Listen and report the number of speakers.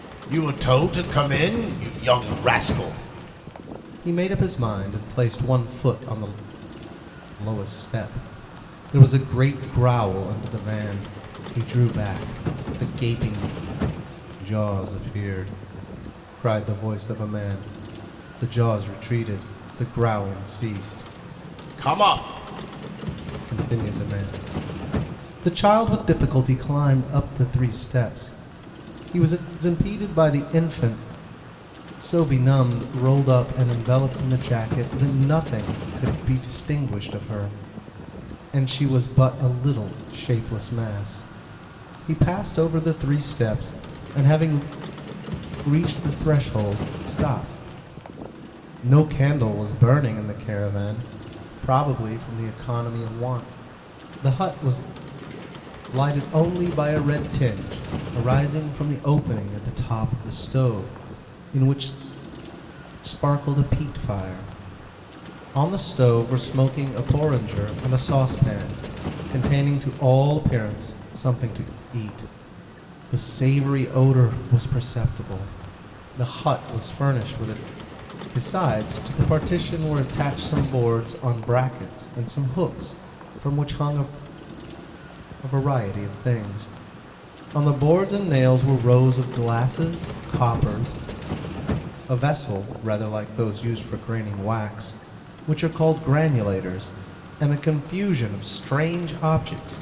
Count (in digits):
1